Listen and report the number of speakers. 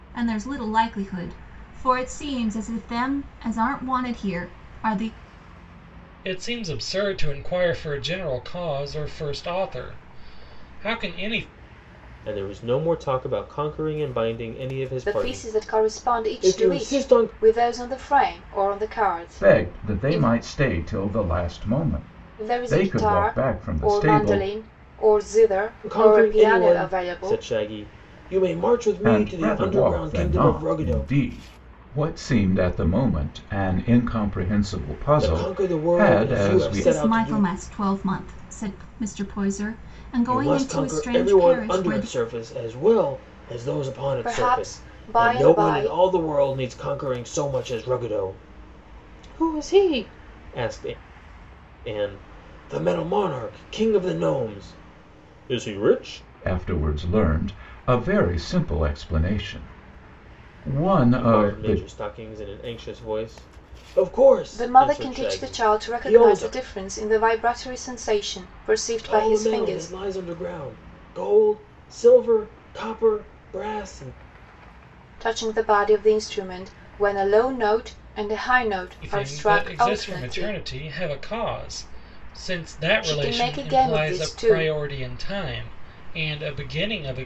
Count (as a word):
five